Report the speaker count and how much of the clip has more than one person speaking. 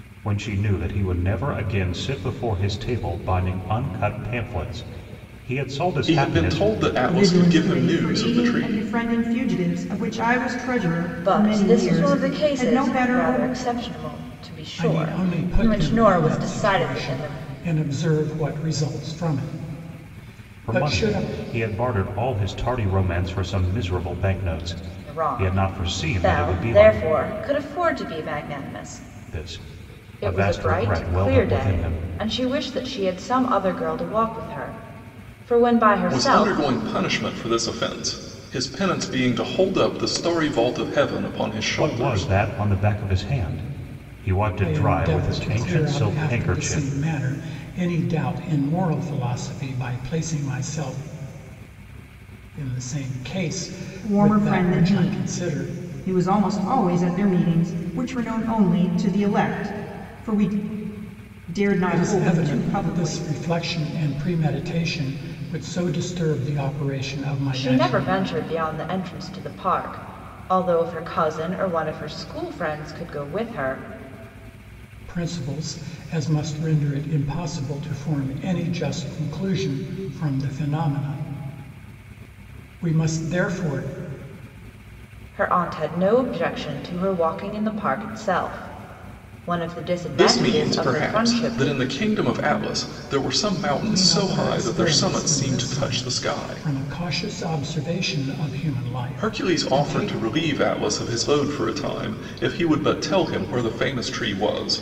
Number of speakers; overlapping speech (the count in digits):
5, about 24%